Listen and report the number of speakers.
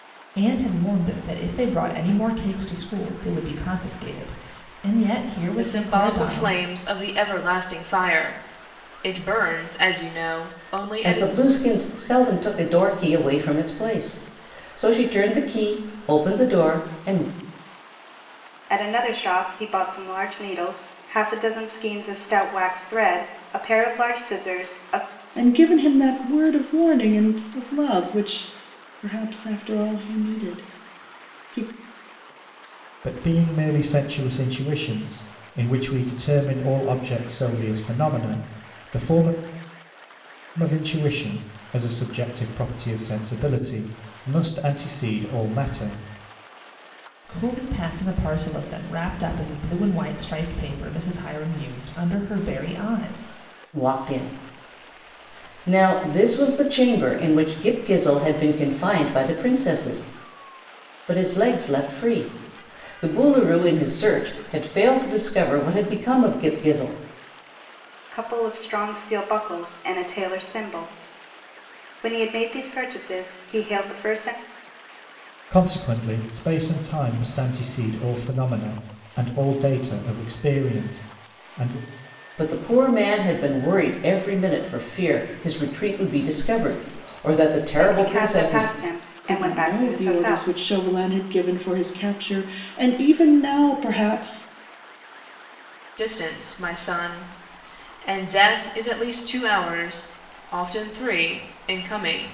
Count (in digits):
6